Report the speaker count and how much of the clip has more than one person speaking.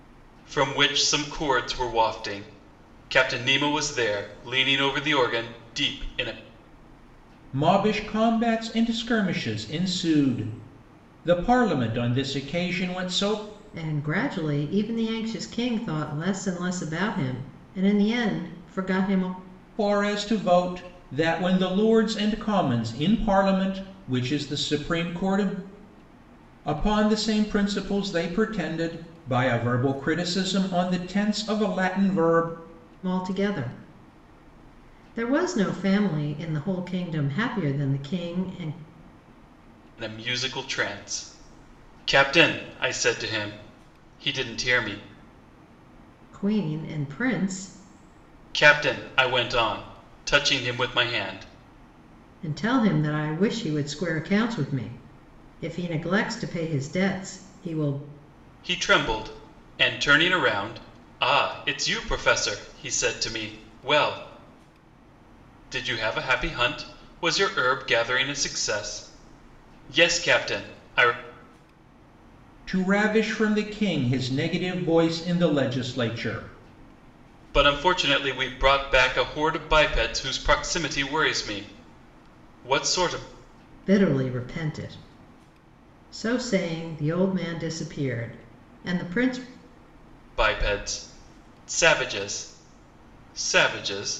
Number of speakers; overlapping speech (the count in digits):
3, no overlap